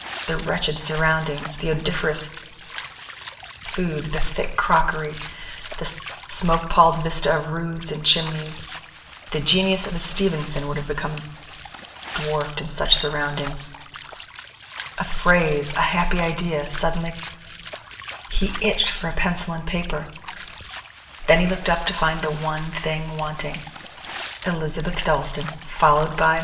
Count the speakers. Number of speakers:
one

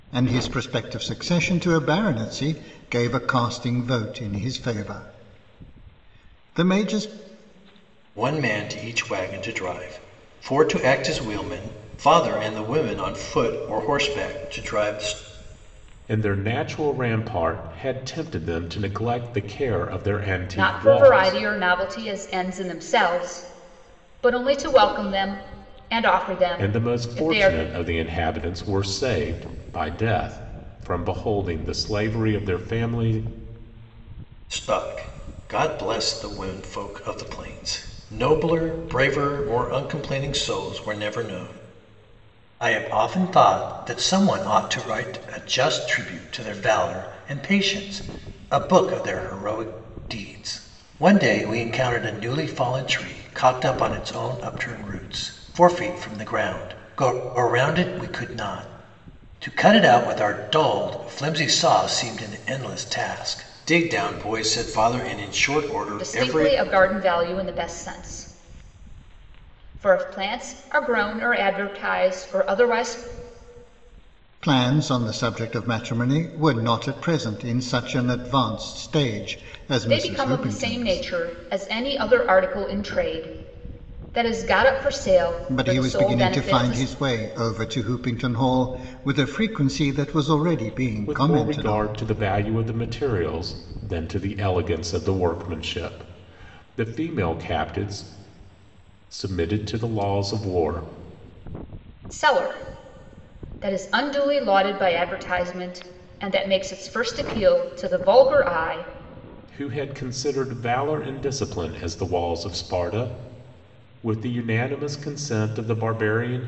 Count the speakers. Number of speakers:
four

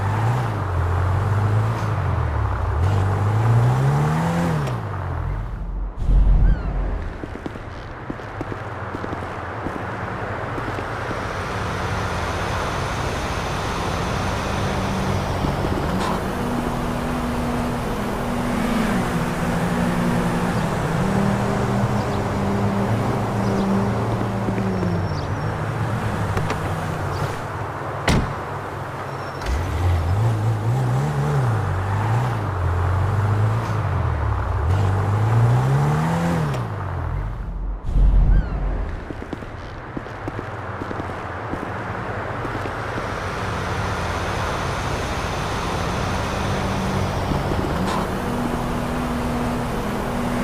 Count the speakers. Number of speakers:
zero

